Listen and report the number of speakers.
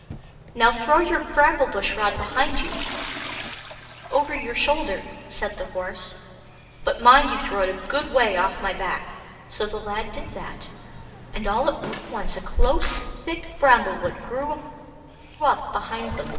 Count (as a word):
one